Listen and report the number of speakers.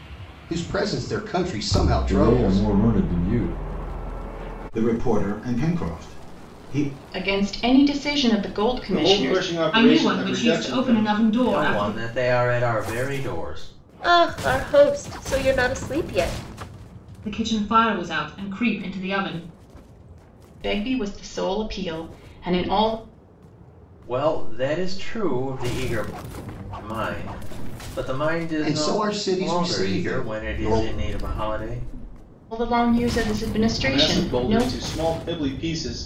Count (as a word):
eight